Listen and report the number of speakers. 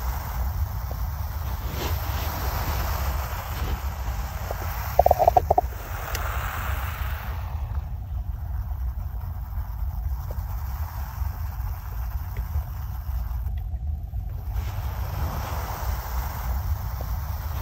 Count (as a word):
zero